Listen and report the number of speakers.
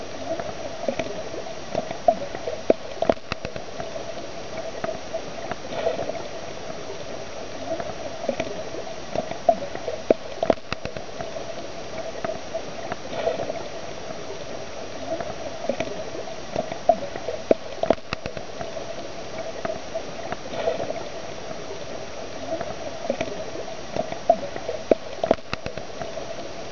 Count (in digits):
0